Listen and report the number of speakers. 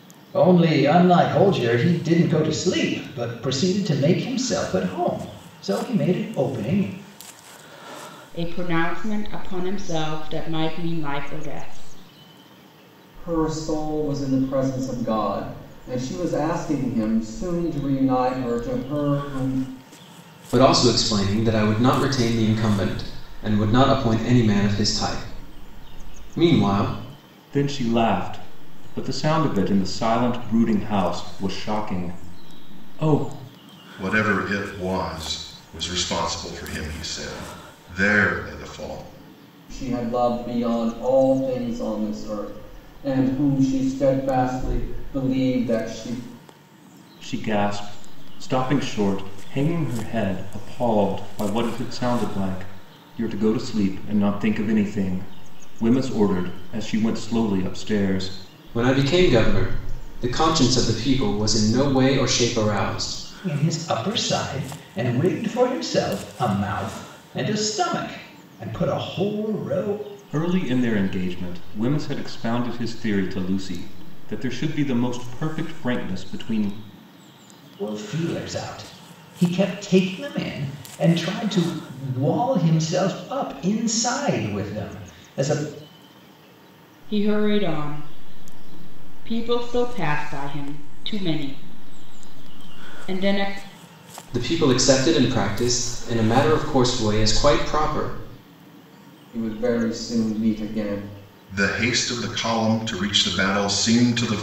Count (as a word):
six